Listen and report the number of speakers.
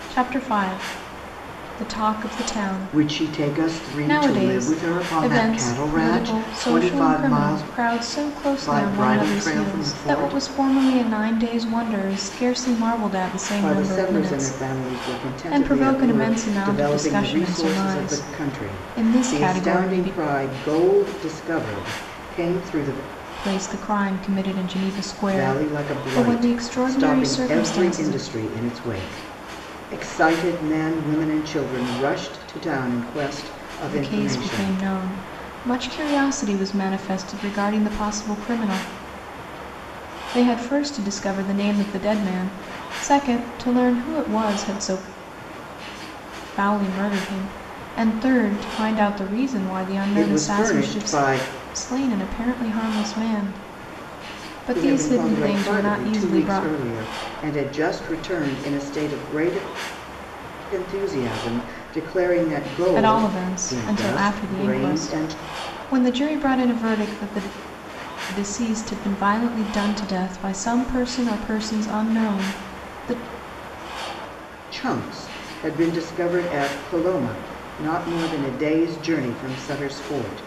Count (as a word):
two